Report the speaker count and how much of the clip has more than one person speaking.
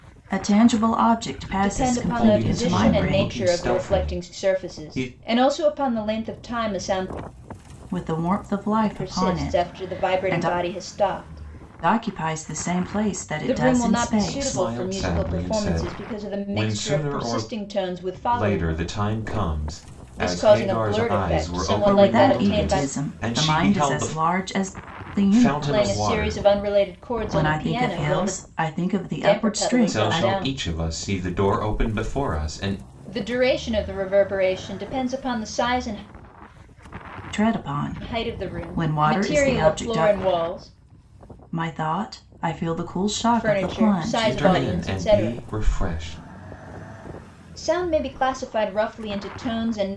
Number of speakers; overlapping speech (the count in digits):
3, about 44%